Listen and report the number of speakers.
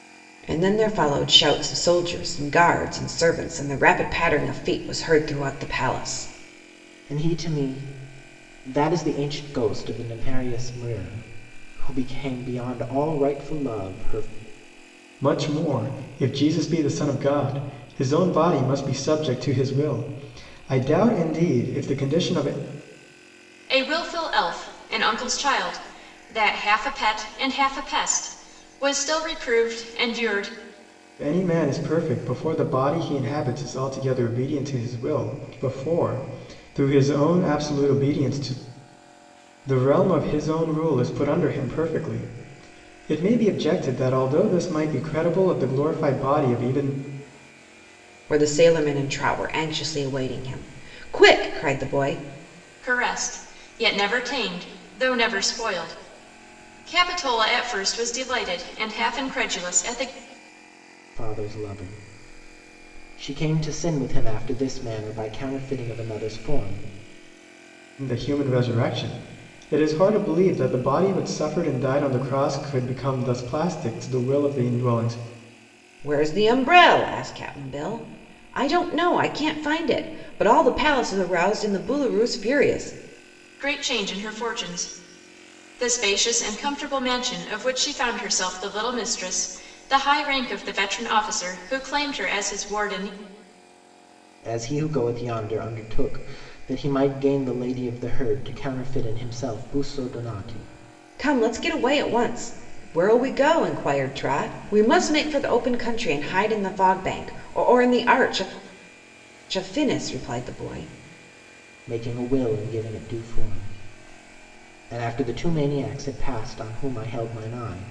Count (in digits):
4